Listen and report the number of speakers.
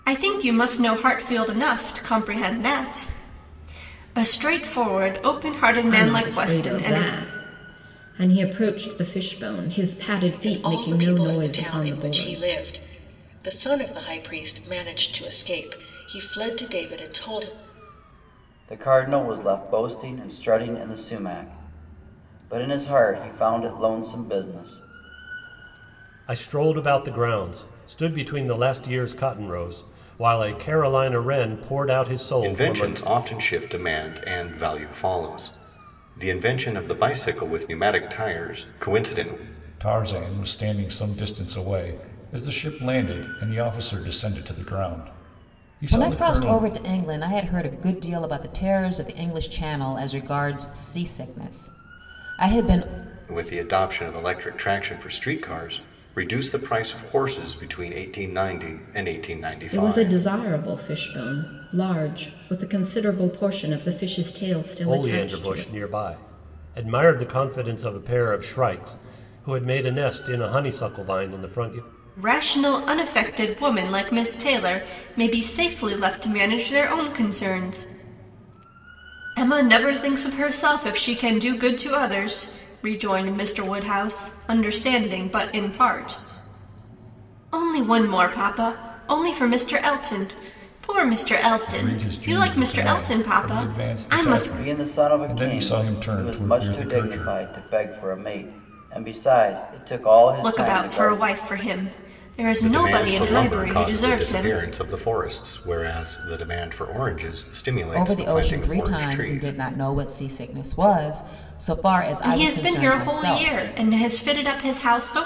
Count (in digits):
8